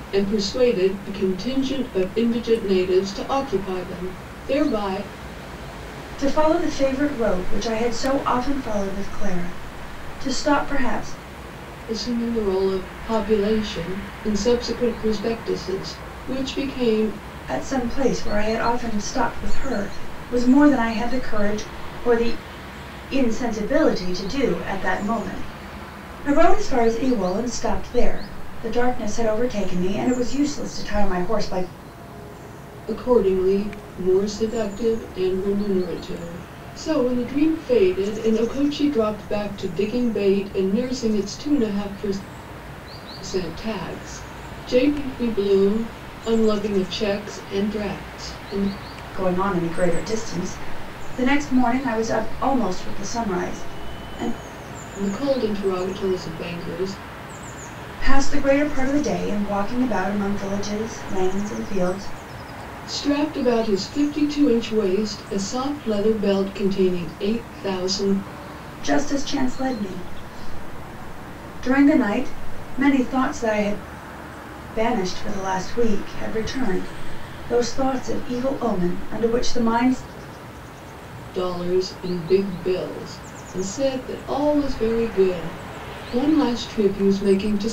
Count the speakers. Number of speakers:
two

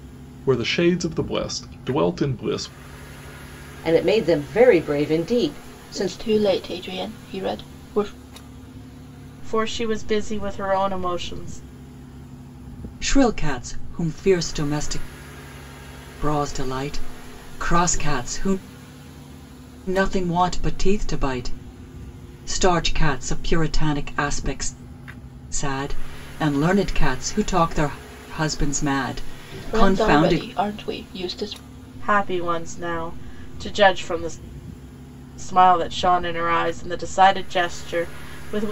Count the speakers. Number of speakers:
five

